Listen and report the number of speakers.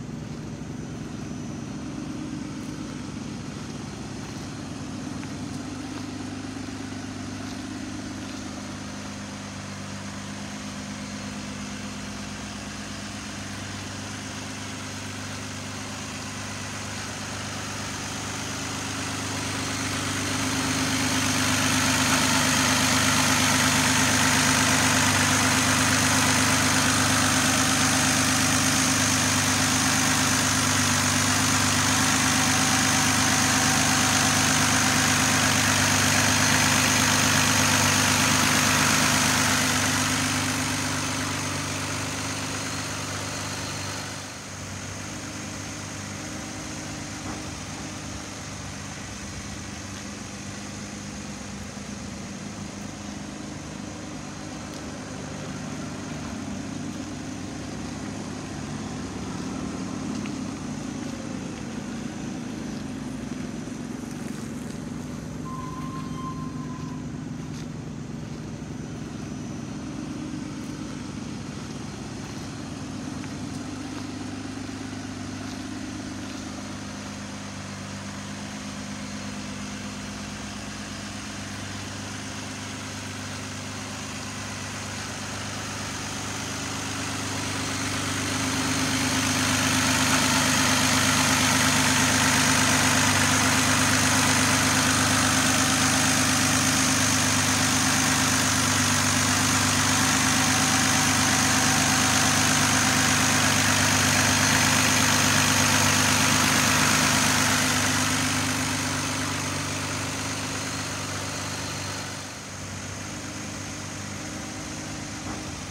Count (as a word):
zero